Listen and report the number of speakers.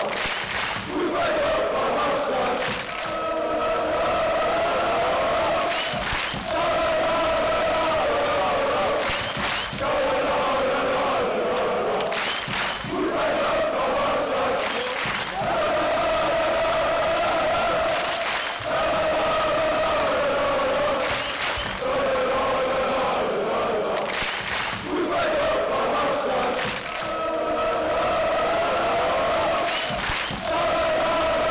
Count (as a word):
zero